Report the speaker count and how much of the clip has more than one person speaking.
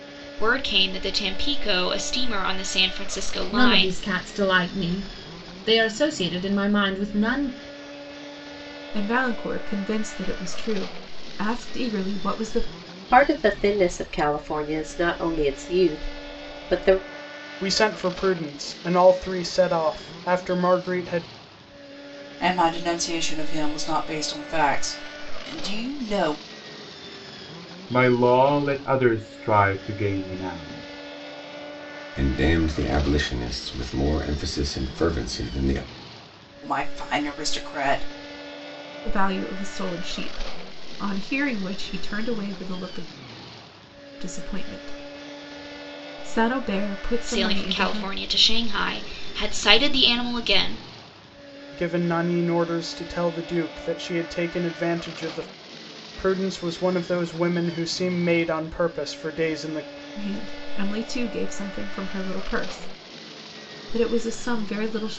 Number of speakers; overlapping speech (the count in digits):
8, about 2%